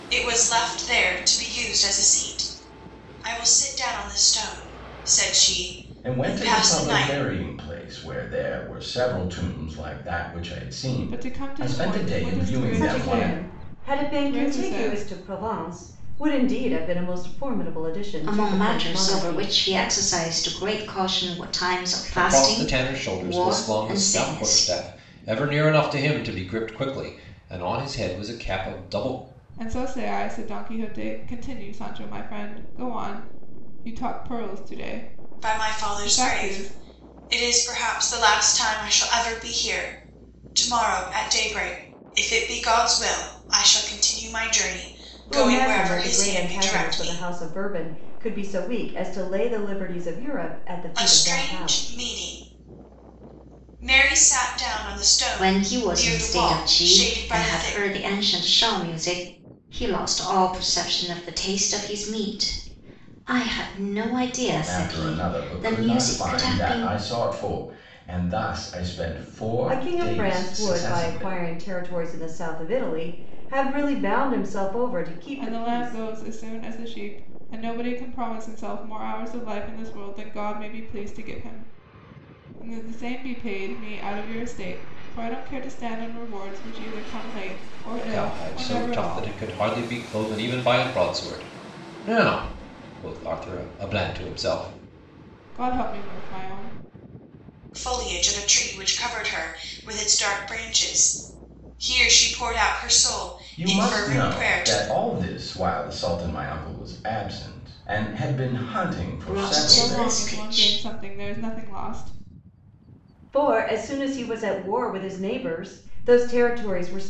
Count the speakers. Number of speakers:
6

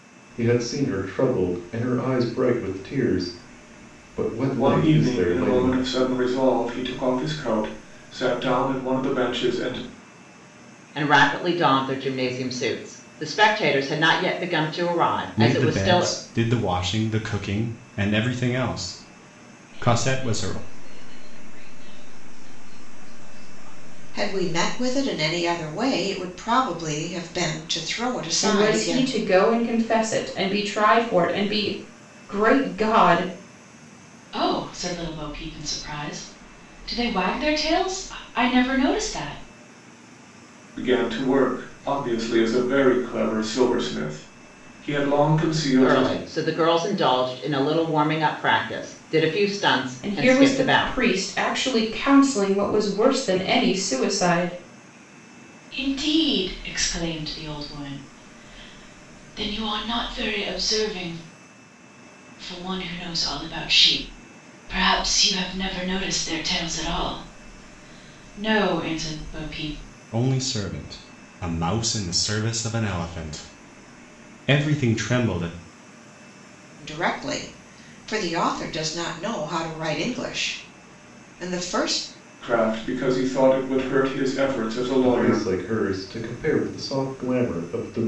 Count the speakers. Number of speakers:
8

